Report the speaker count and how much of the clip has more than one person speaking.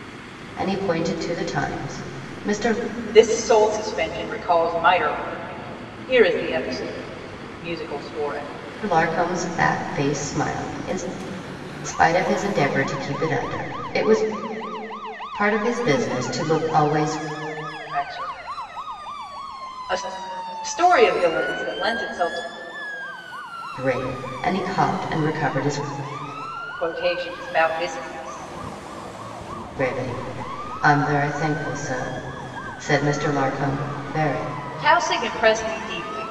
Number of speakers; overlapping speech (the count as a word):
two, no overlap